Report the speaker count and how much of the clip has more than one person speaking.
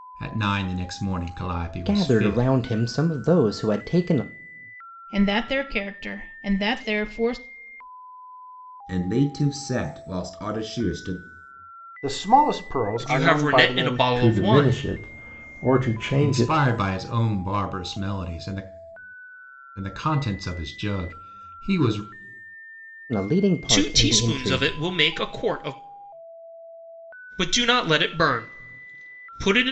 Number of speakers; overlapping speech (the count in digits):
7, about 14%